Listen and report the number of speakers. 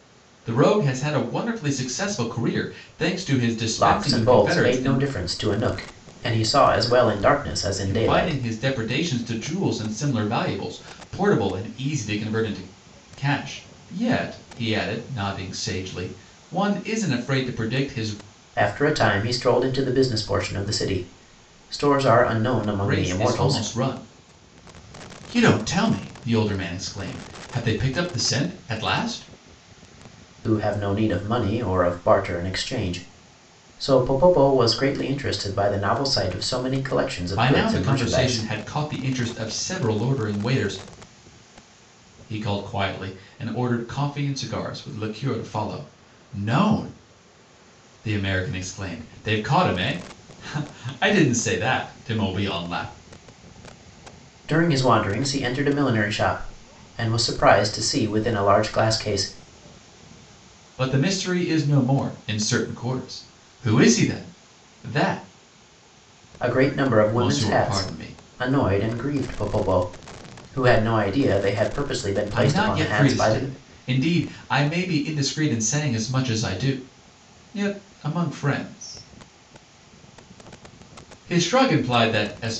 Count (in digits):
2